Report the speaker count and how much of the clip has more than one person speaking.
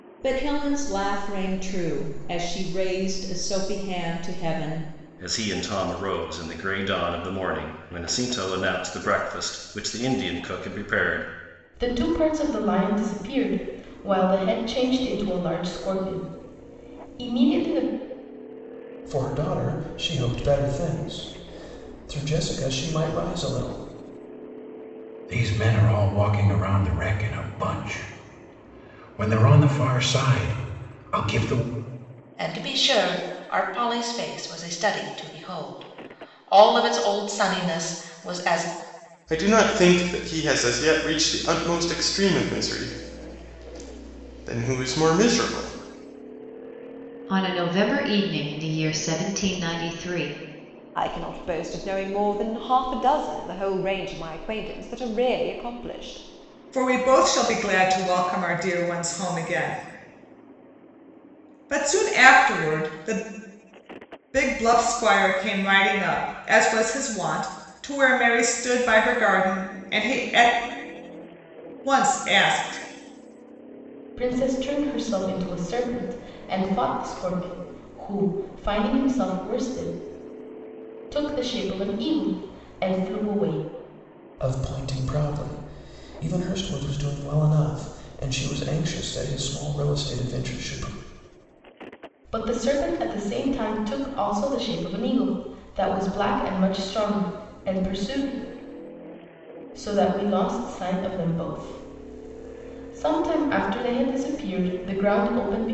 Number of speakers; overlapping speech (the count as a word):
ten, no overlap